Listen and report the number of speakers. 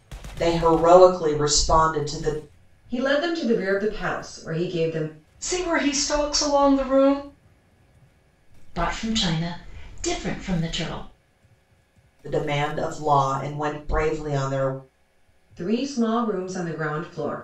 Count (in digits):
4